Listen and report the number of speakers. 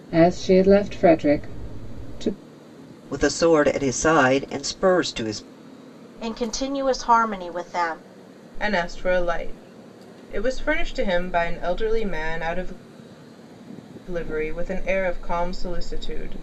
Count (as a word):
four